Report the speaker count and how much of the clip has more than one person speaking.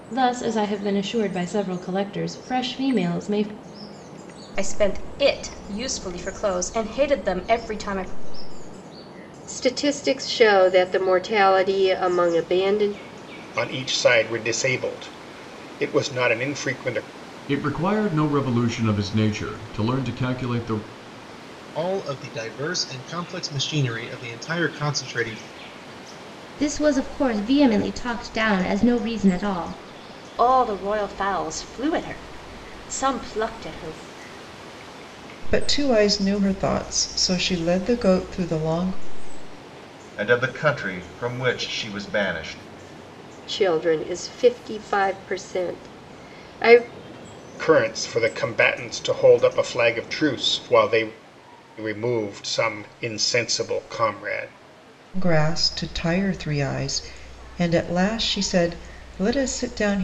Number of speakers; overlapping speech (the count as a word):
ten, no overlap